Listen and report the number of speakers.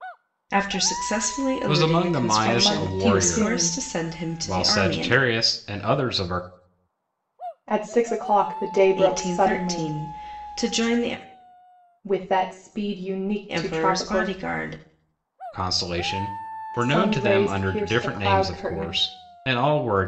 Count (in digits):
3